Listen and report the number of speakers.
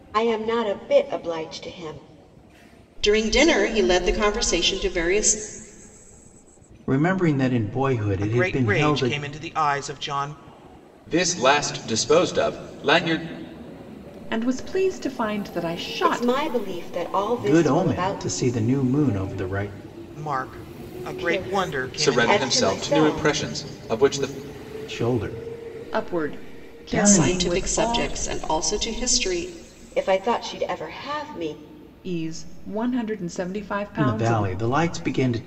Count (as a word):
six